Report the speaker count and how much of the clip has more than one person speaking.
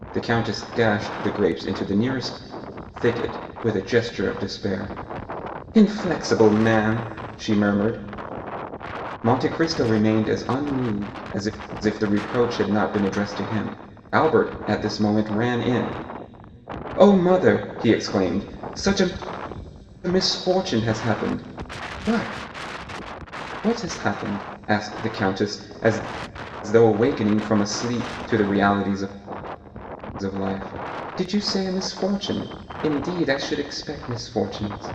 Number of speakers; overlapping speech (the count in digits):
1, no overlap